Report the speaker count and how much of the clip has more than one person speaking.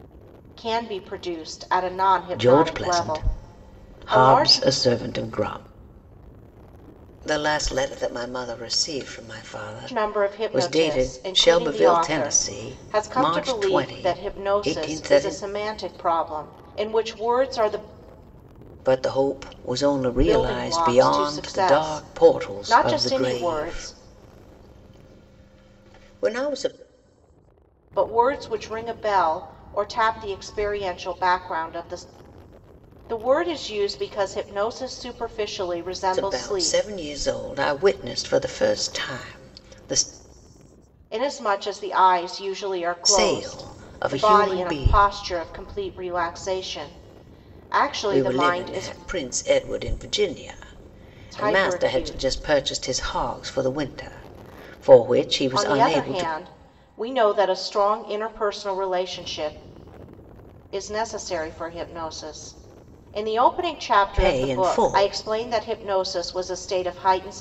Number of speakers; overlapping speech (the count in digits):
2, about 27%